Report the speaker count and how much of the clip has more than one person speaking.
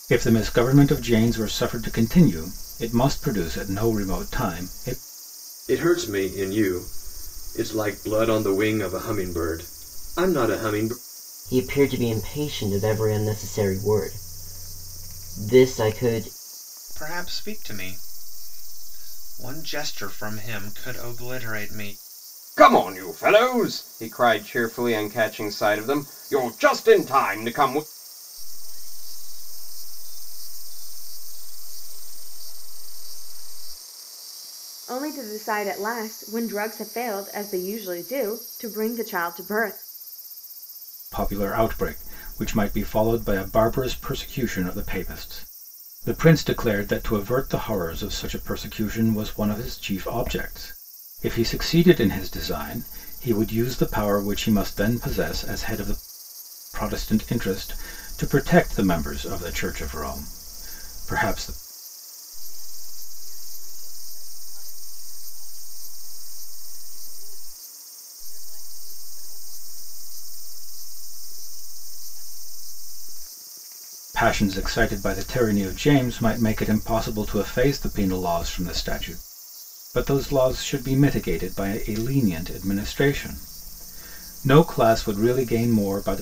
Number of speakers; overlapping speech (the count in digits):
7, no overlap